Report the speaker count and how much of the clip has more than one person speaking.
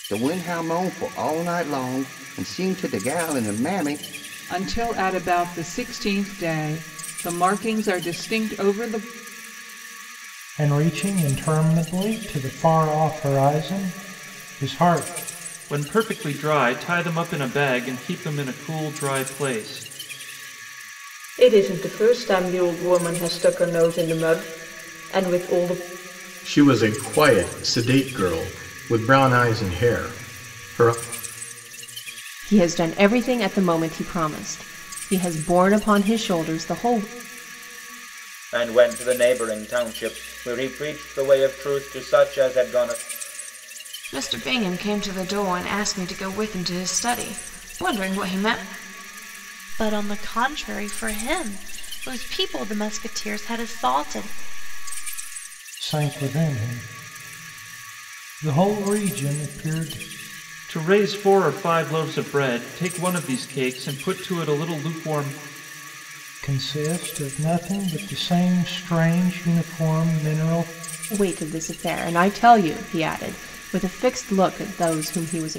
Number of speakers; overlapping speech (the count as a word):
ten, no overlap